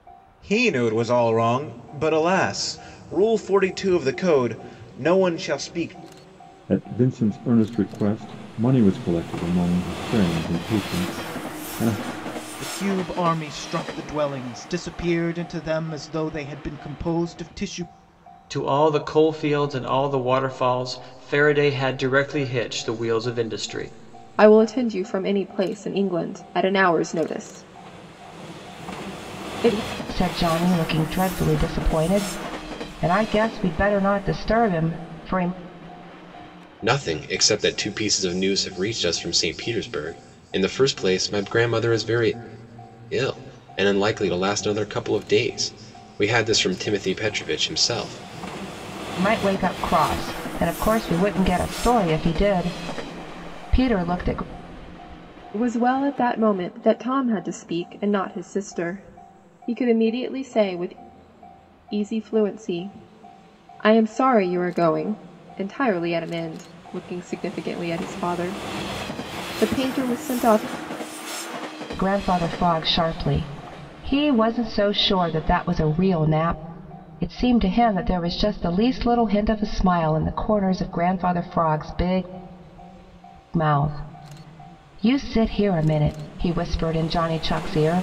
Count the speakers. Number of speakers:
seven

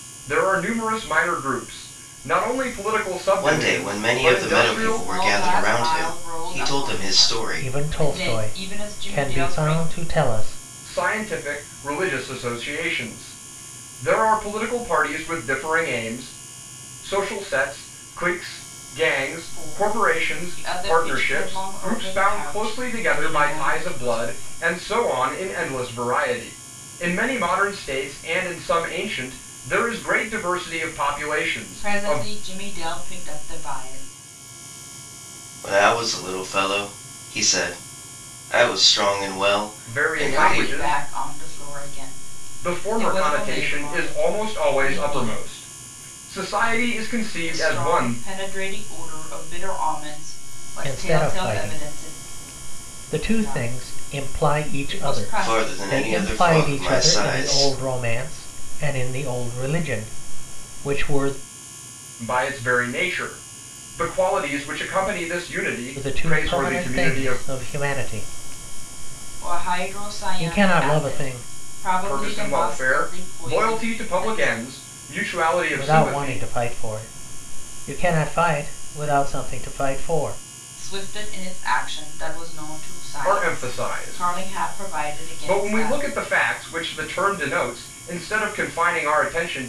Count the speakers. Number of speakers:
four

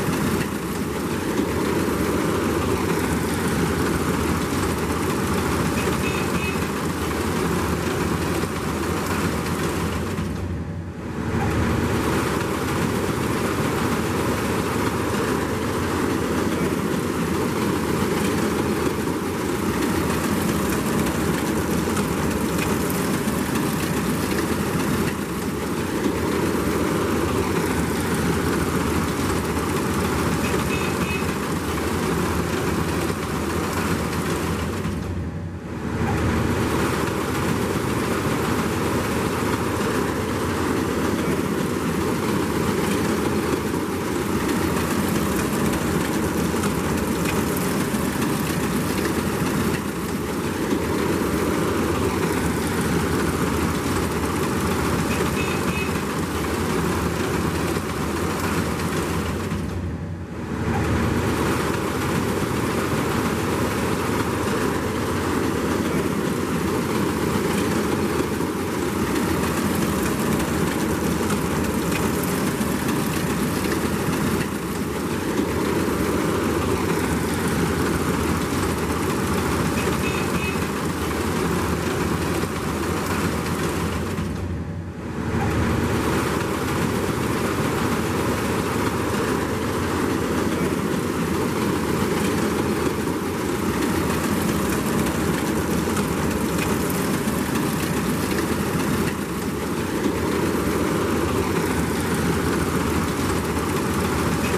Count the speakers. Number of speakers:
zero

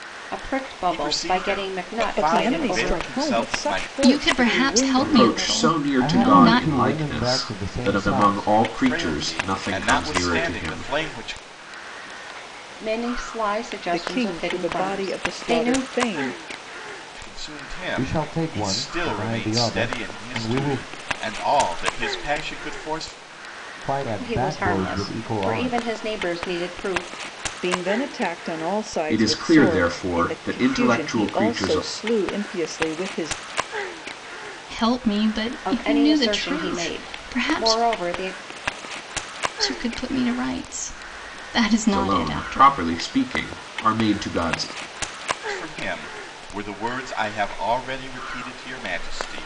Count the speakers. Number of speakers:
six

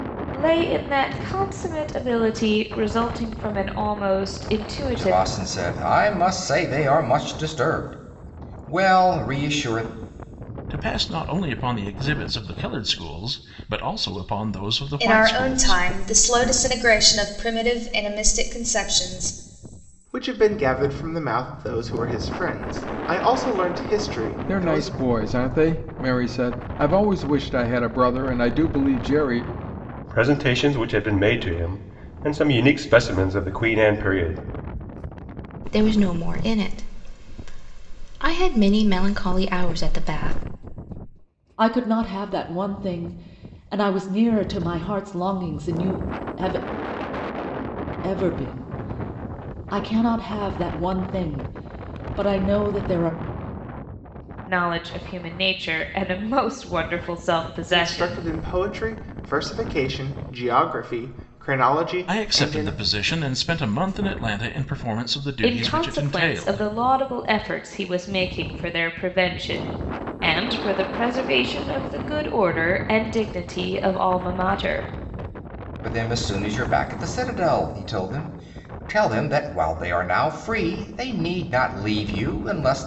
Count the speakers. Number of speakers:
nine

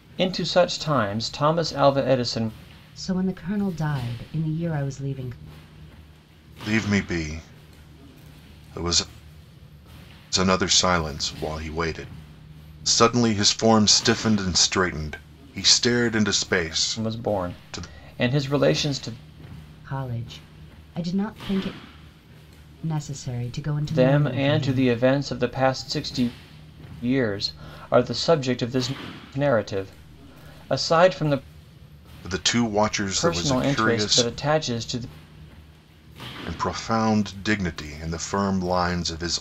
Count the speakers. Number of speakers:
three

